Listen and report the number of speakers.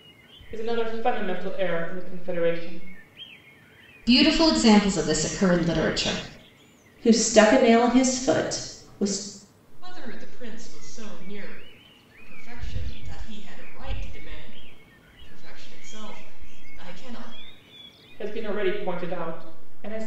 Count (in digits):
4